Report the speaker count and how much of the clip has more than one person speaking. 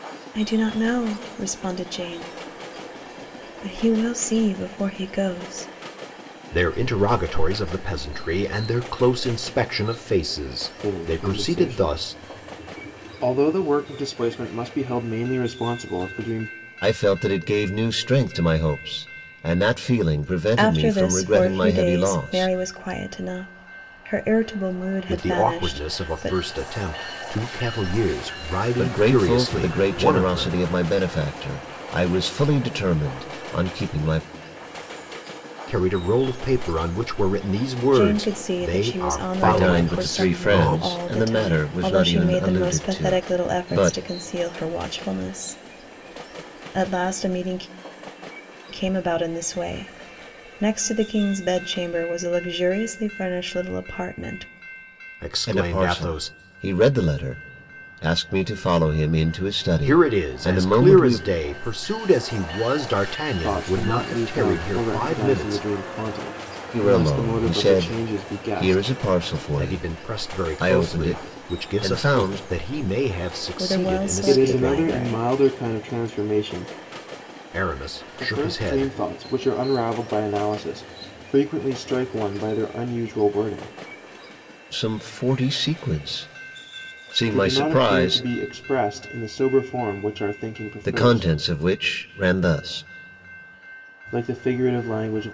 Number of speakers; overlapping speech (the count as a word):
four, about 28%